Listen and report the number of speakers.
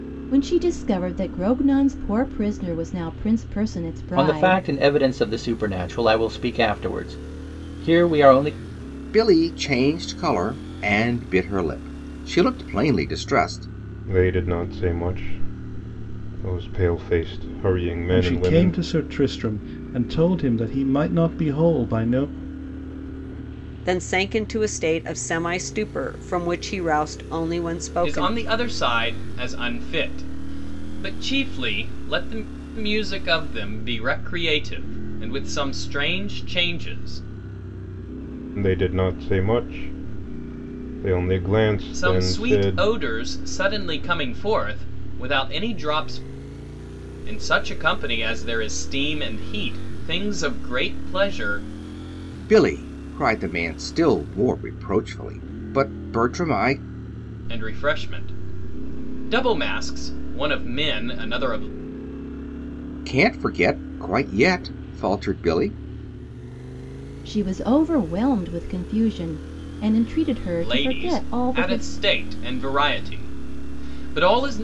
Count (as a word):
seven